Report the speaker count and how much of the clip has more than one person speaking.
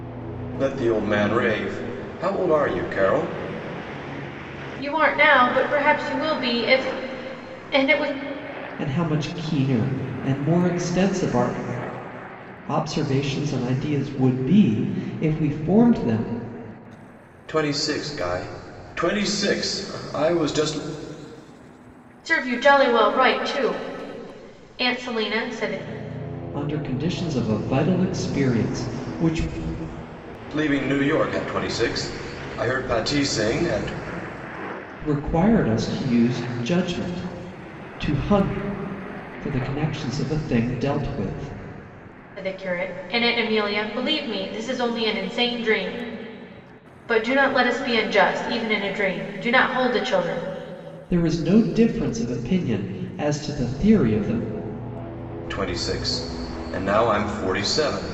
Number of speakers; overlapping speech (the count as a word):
three, no overlap